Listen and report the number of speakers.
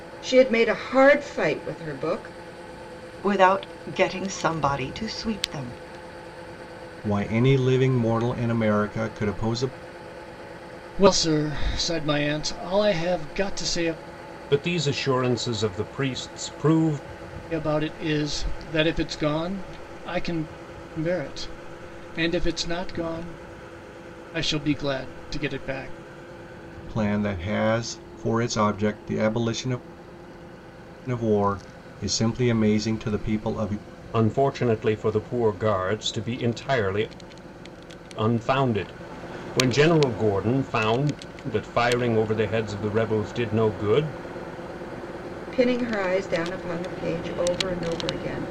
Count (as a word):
five